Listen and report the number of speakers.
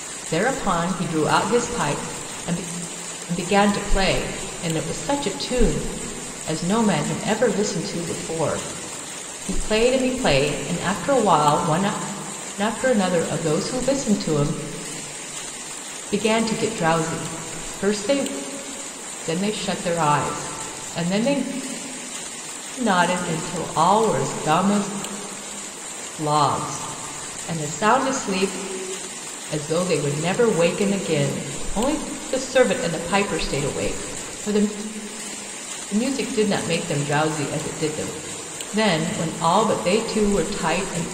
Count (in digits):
1